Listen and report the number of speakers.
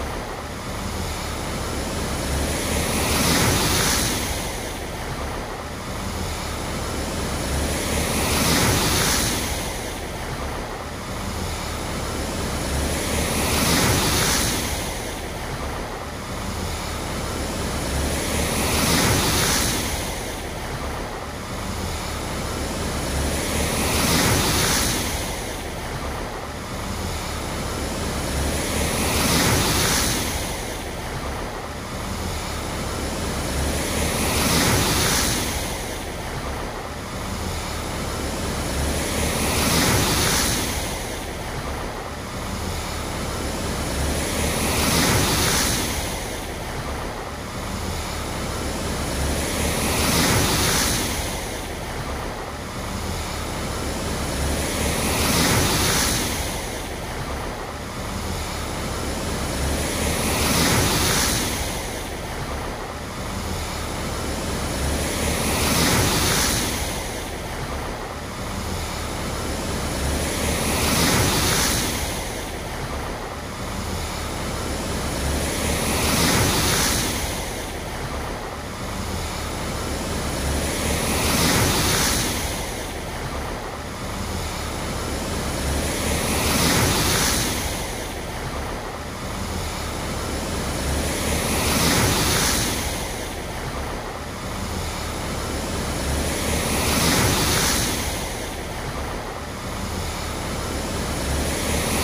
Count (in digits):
0